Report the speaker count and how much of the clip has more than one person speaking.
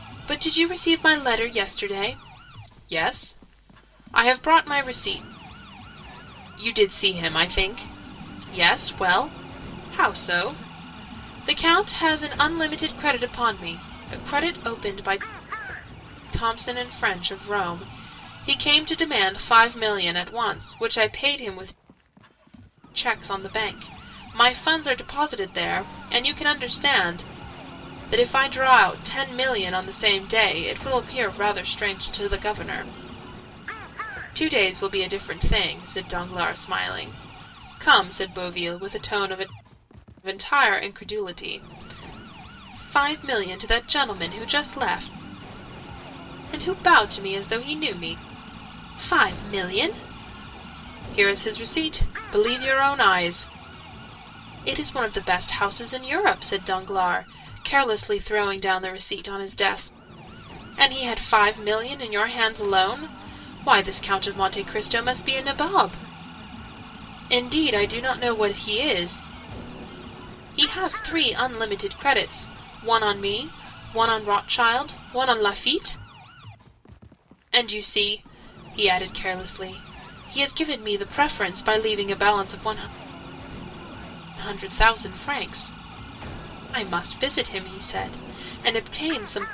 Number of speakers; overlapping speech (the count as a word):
one, no overlap